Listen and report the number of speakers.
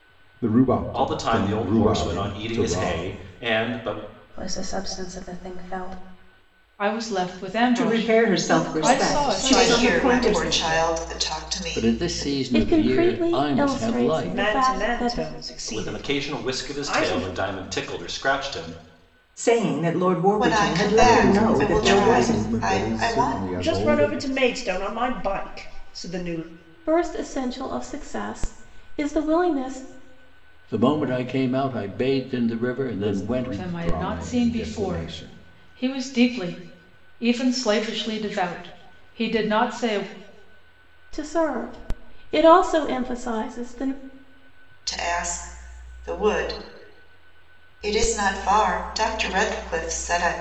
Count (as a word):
nine